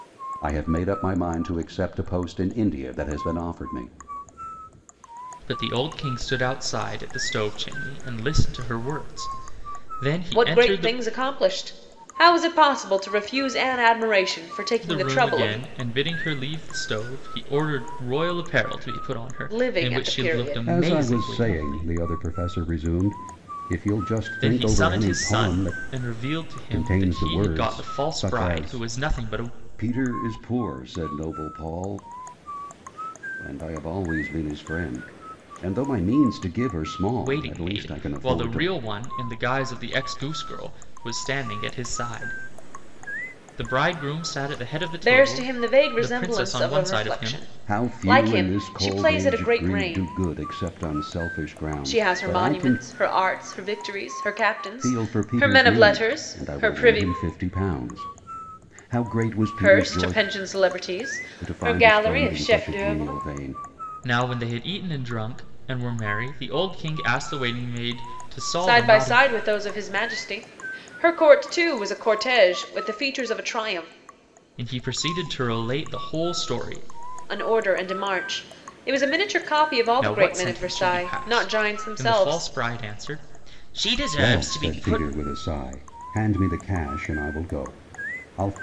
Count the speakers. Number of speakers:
3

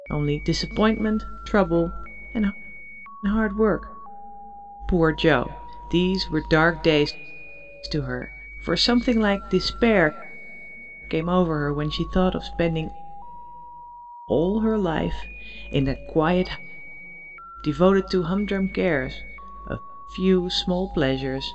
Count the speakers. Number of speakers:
1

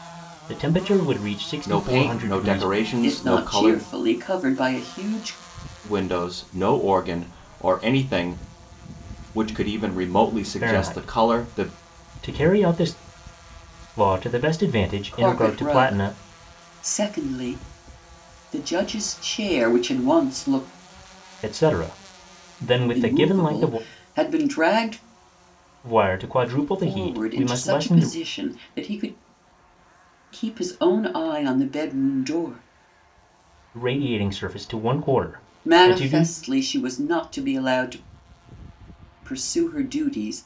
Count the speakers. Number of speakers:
3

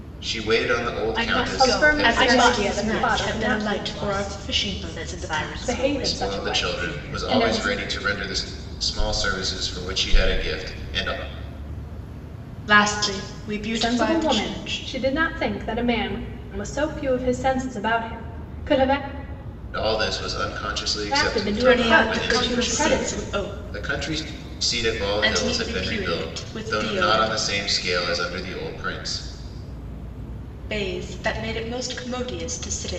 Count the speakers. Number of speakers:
4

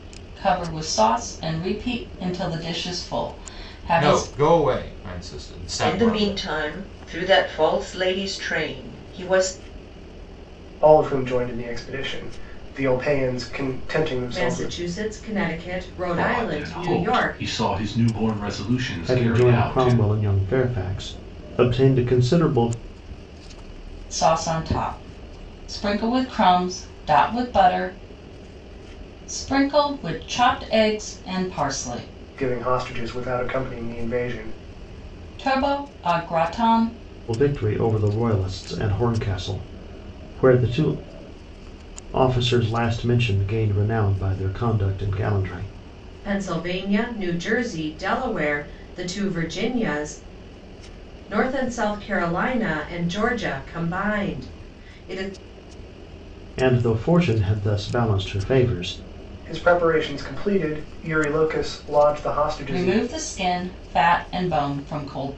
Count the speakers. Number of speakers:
7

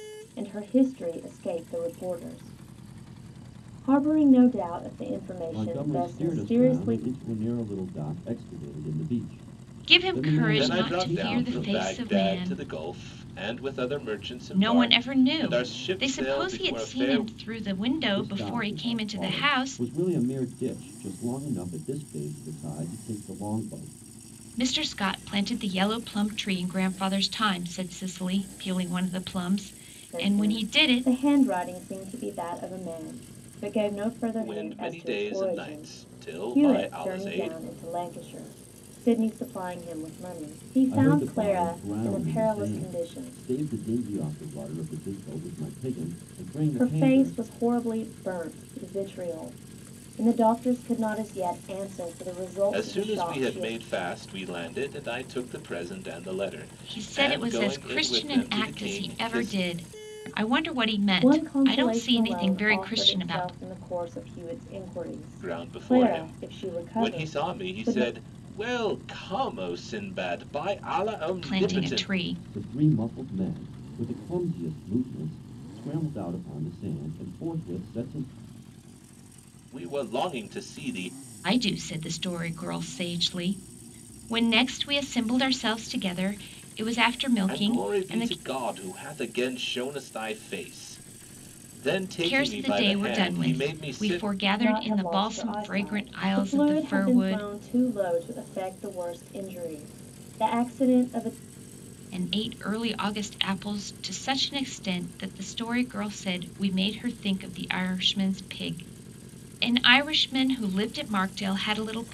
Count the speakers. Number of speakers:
4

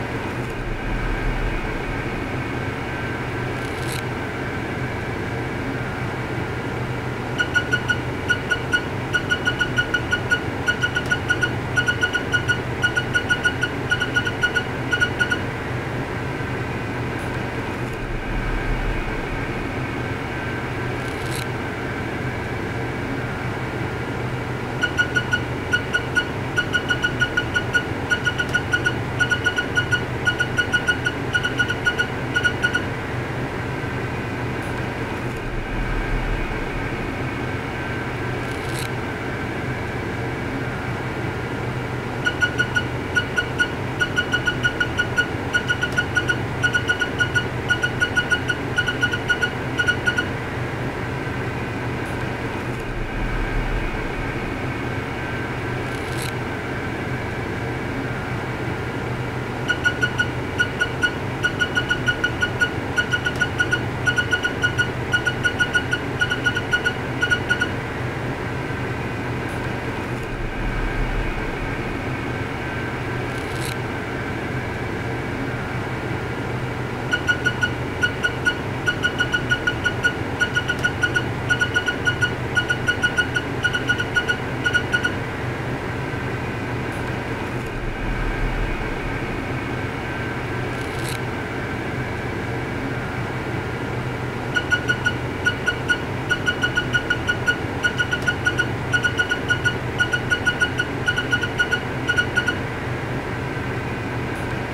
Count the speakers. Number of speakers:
0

